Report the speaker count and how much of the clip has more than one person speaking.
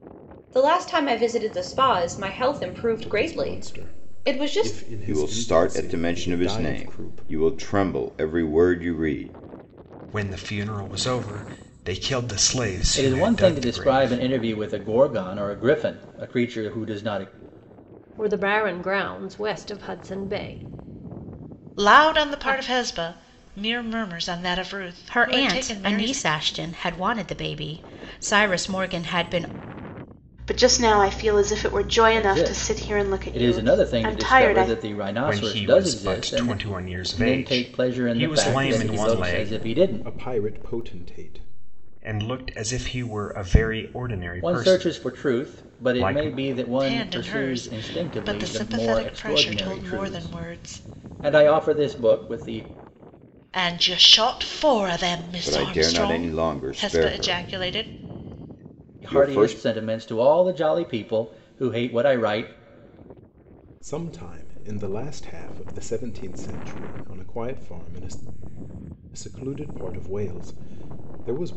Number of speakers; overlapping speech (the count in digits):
9, about 33%